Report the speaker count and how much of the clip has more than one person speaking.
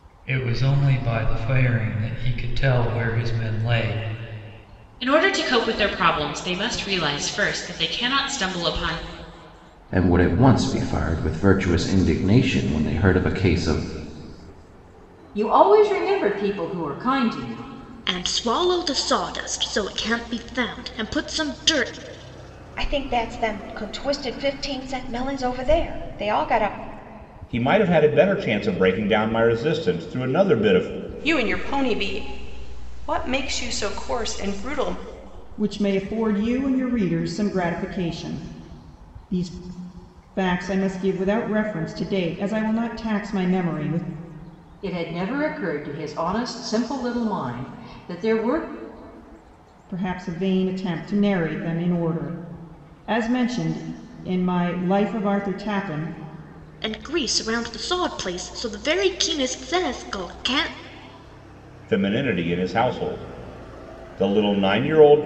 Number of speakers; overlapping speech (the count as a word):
nine, no overlap